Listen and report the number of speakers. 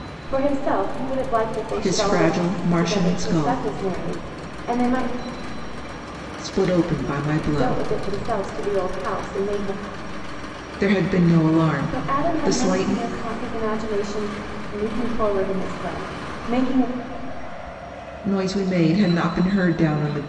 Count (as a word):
two